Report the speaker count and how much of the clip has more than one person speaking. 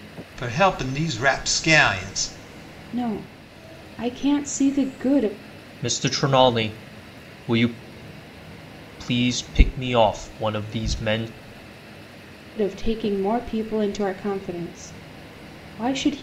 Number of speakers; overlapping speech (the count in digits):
3, no overlap